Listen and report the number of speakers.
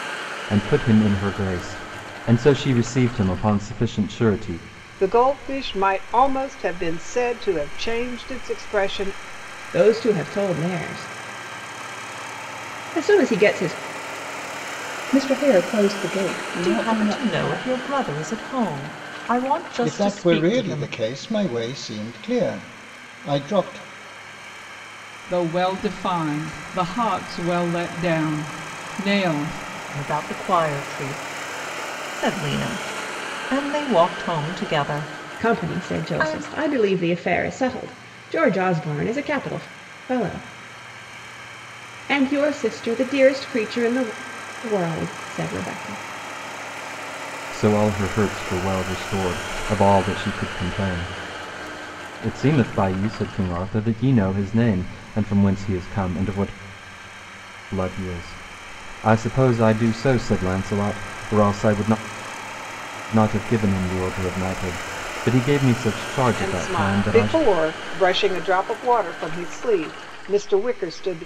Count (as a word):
seven